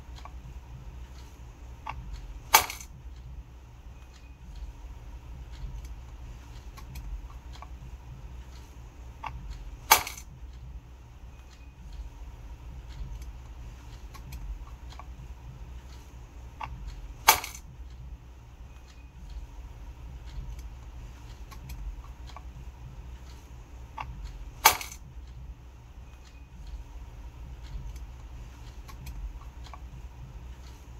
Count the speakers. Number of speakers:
zero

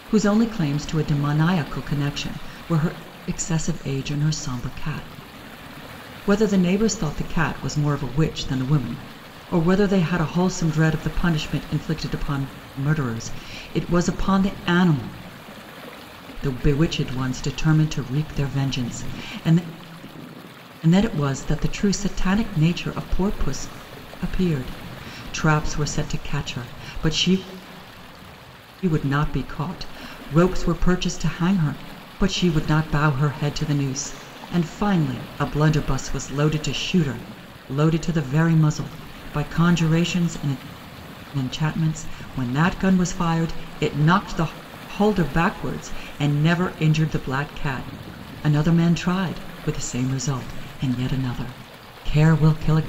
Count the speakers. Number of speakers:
one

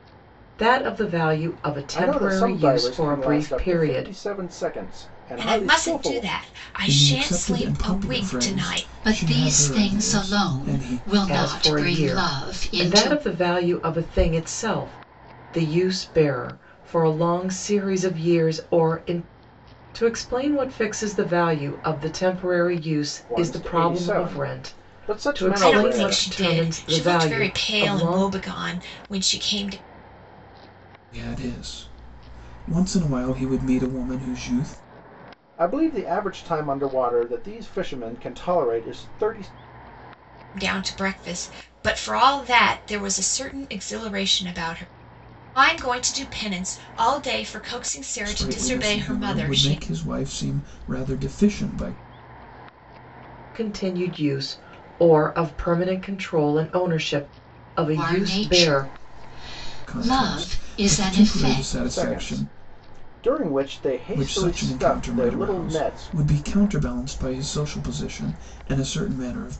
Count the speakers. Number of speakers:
five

